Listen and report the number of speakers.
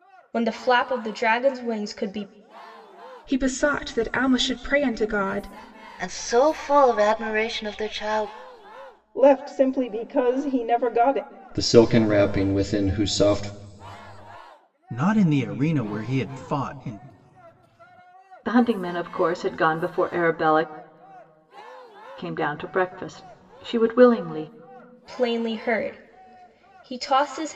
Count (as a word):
seven